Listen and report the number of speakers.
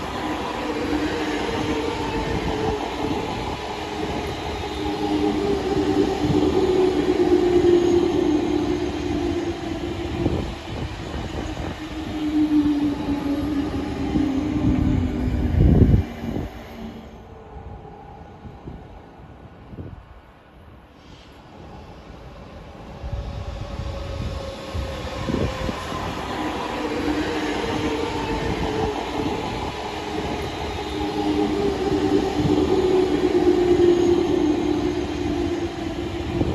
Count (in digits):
0